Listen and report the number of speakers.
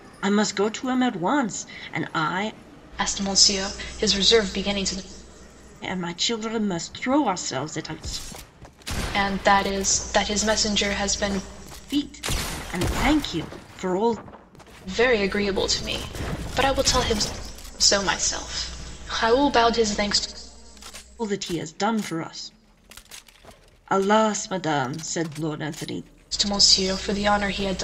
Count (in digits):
2